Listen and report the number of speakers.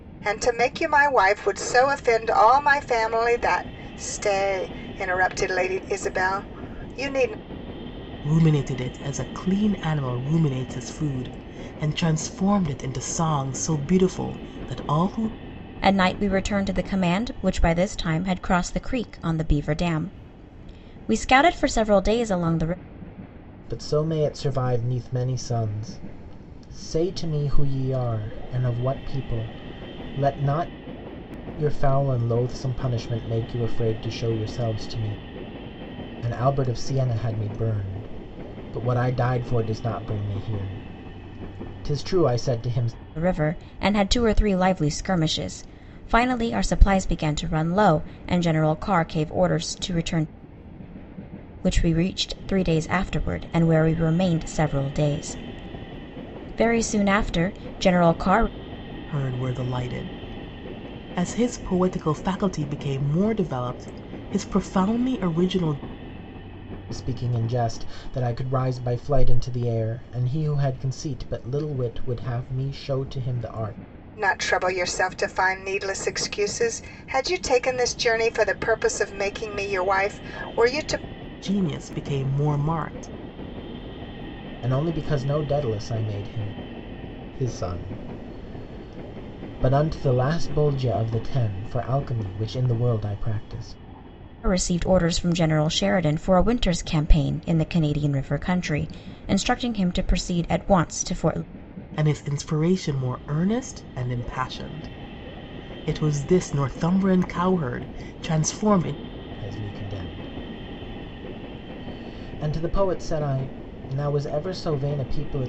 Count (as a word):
four